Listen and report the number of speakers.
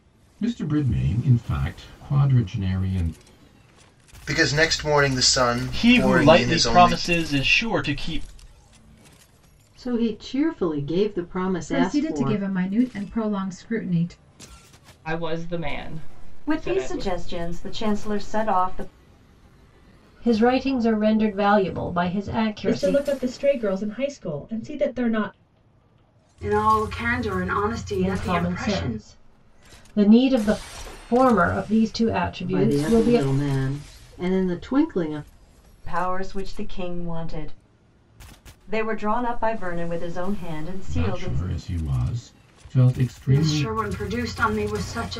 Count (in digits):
10